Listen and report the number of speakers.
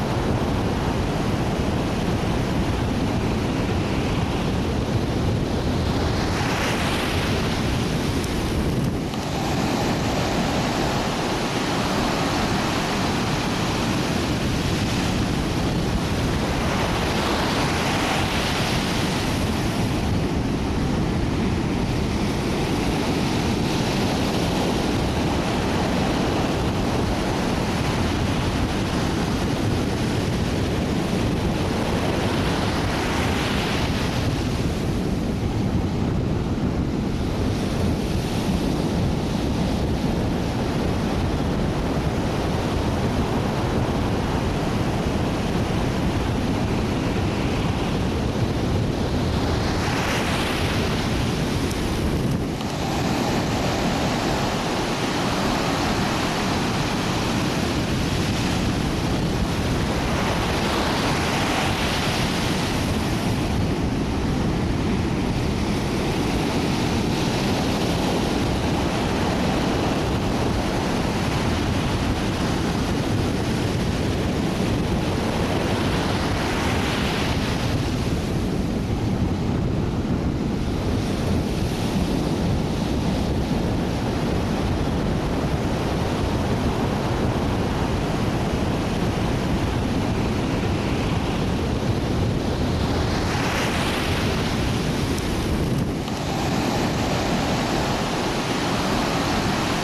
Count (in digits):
0